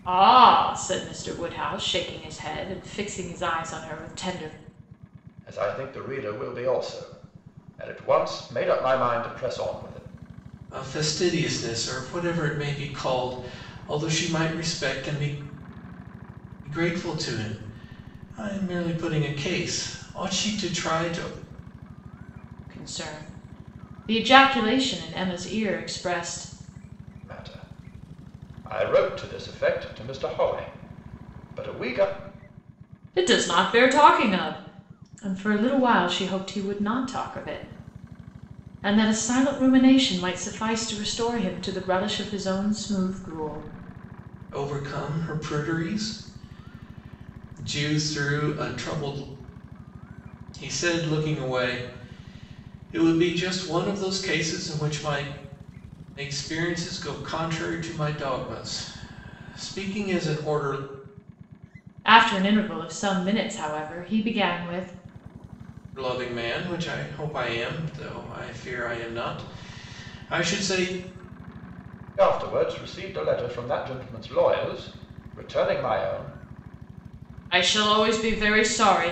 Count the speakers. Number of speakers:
three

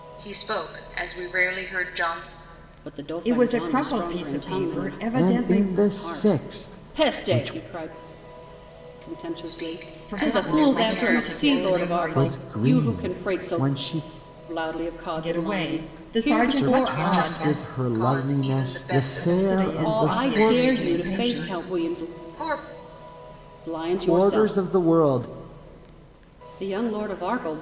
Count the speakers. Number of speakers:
four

